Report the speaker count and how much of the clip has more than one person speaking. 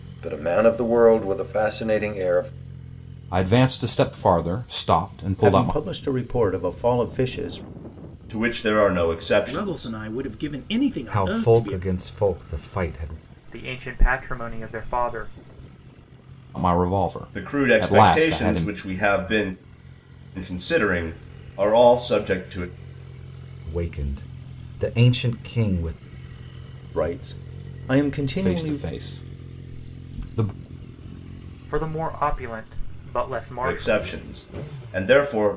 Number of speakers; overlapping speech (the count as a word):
seven, about 11%